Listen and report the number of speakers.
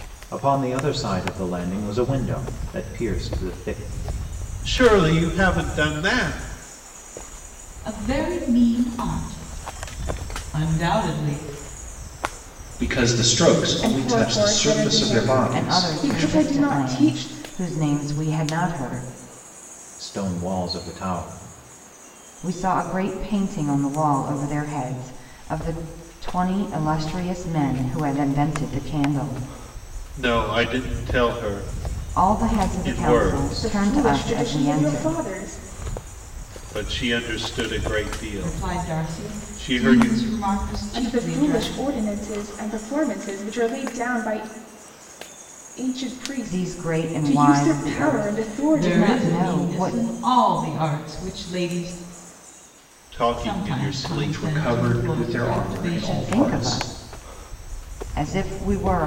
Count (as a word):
six